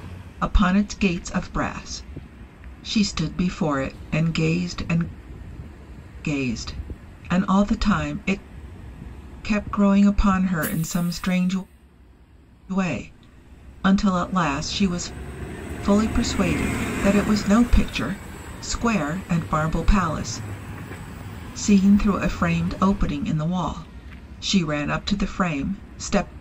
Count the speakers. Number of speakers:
one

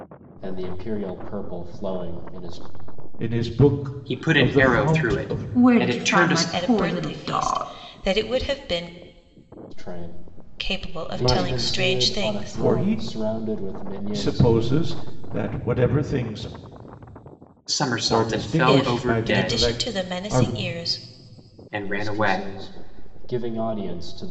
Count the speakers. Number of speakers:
five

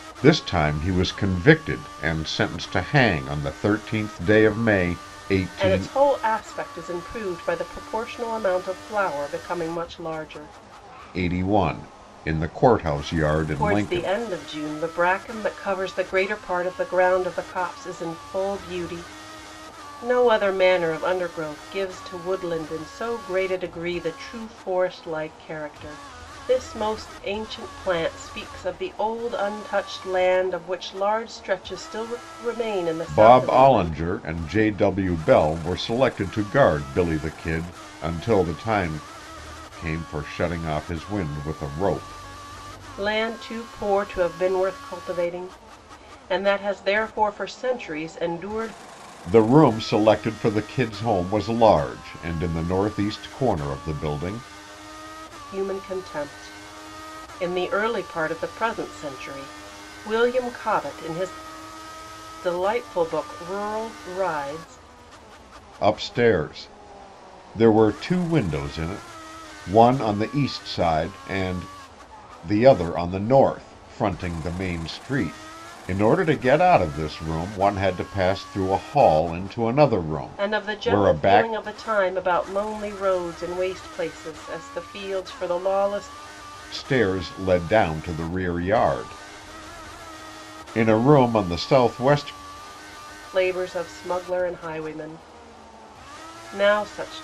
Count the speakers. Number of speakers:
two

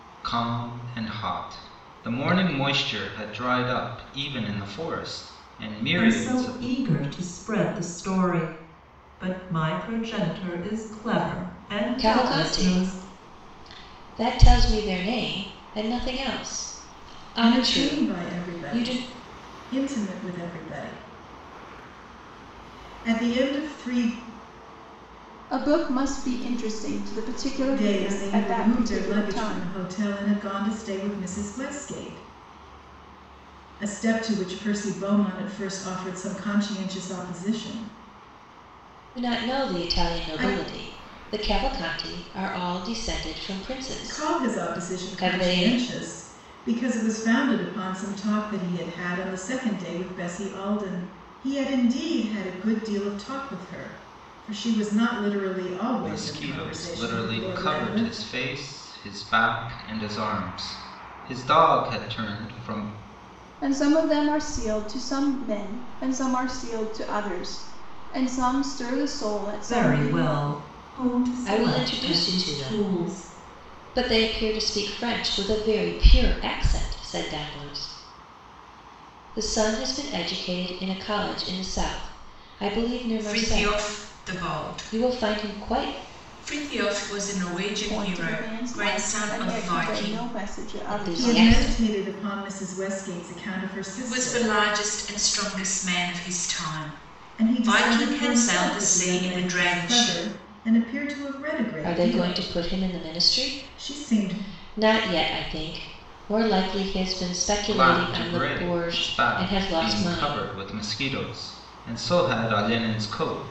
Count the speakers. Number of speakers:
five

